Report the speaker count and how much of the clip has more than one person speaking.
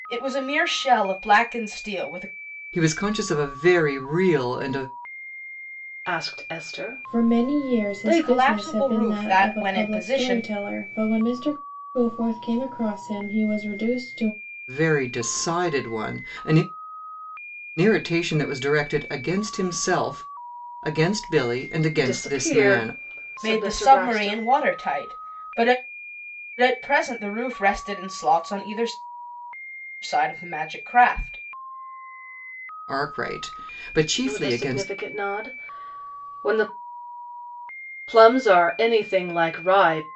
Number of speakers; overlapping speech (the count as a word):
four, about 15%